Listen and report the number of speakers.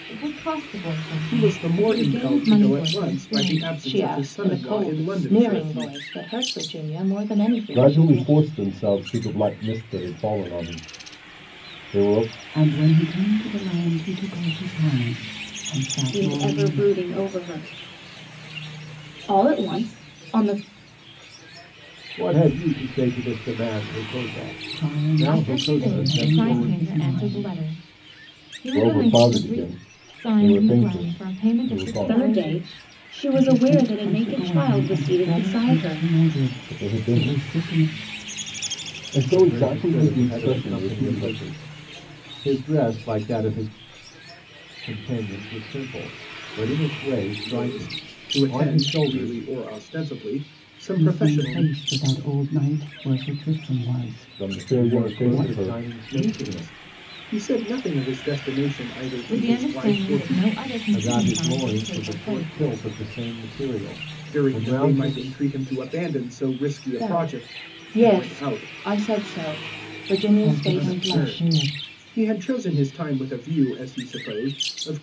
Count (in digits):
7